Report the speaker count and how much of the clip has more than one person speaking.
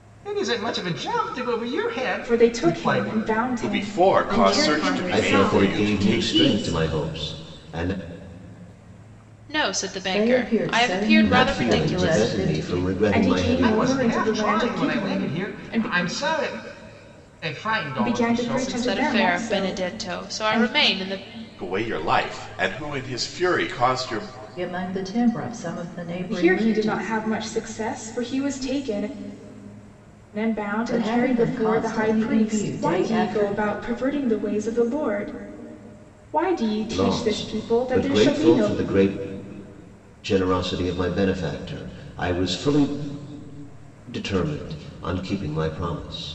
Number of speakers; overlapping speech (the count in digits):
7, about 39%